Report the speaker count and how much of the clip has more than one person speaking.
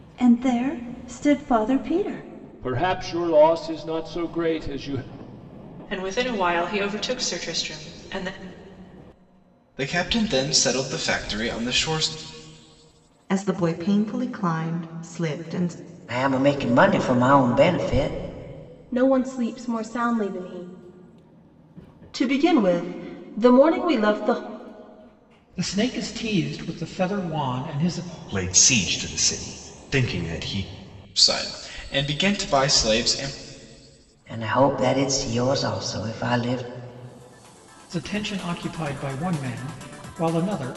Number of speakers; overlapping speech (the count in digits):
10, no overlap